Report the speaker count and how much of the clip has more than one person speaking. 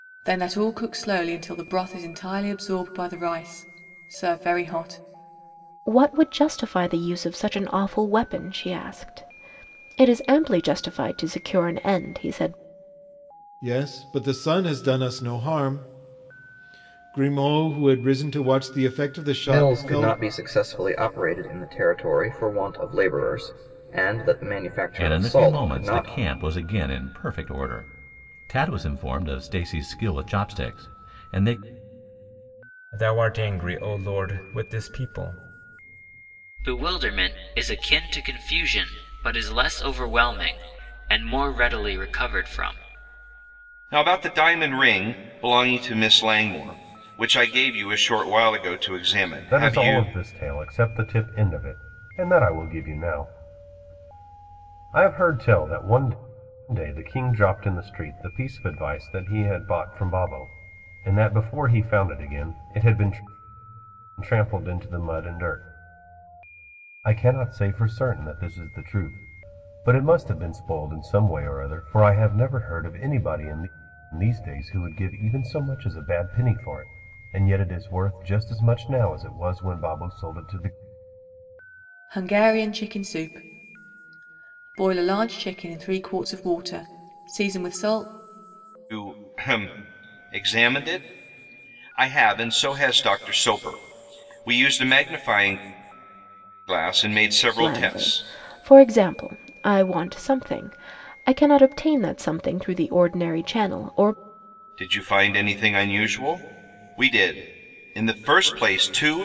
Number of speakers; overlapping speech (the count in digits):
9, about 3%